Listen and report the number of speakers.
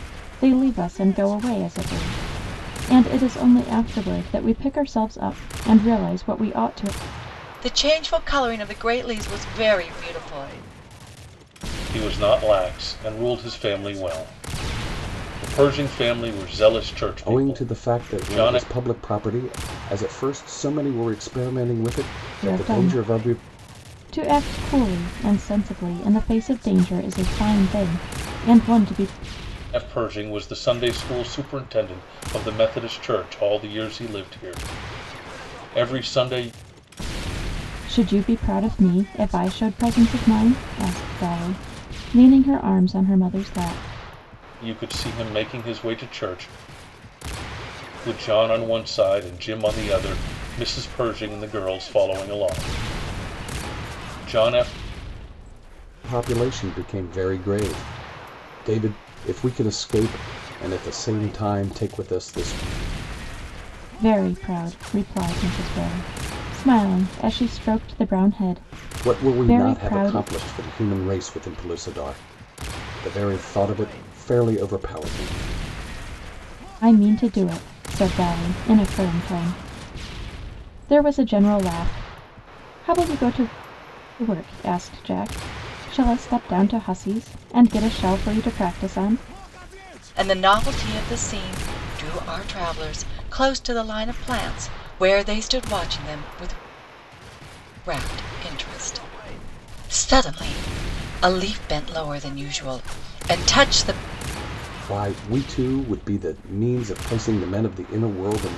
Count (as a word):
four